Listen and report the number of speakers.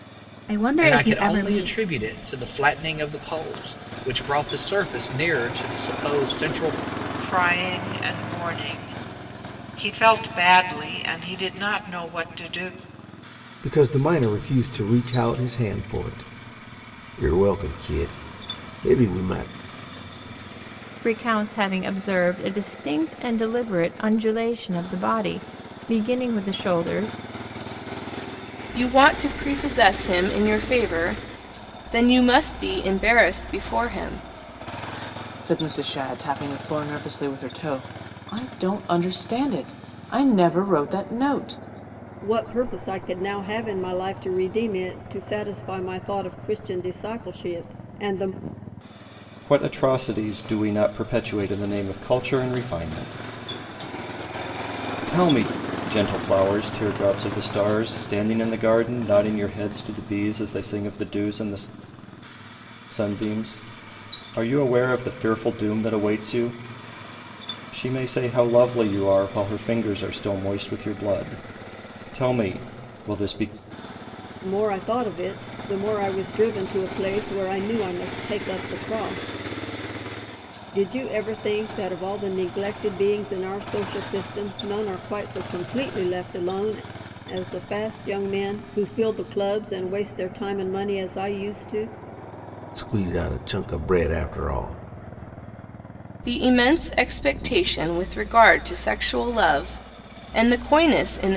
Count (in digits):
9